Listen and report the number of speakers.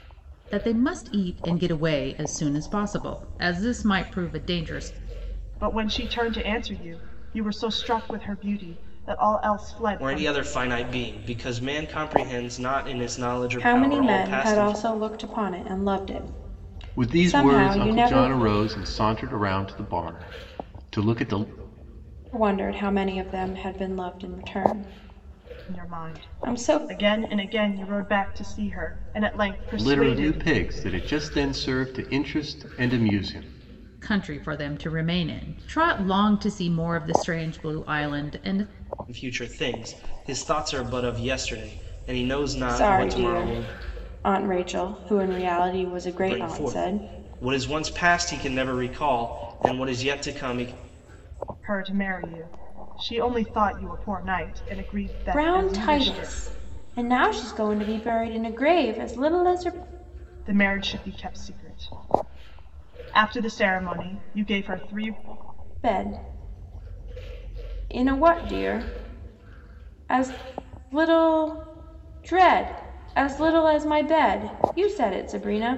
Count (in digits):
5